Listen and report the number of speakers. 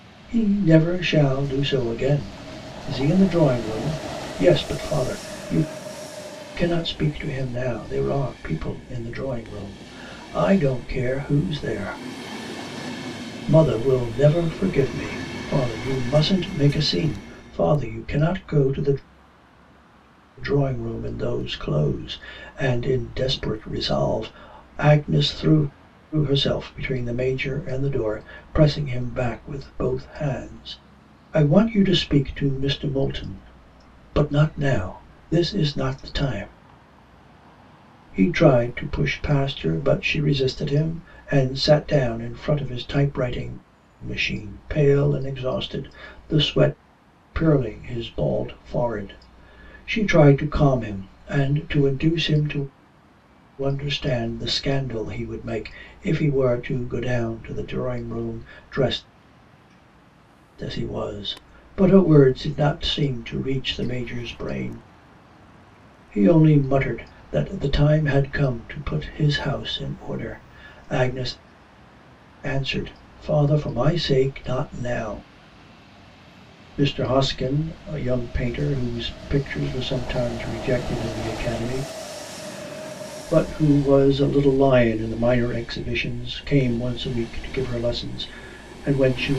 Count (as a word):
one